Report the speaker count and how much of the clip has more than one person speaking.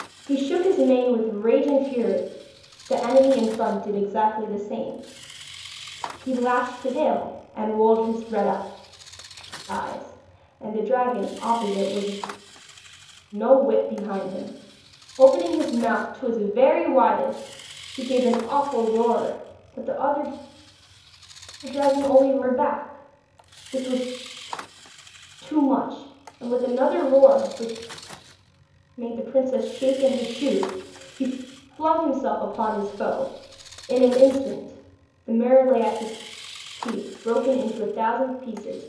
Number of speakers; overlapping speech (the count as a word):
one, no overlap